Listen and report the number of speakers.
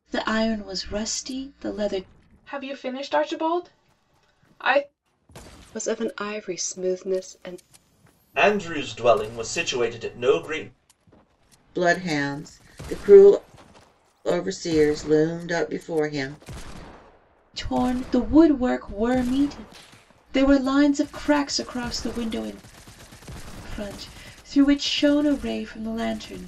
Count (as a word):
five